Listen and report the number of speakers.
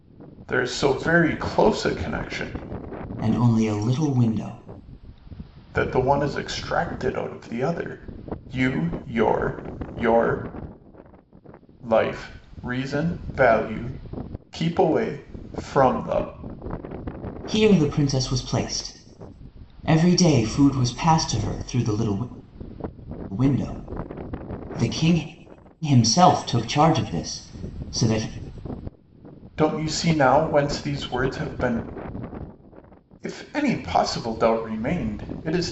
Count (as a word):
two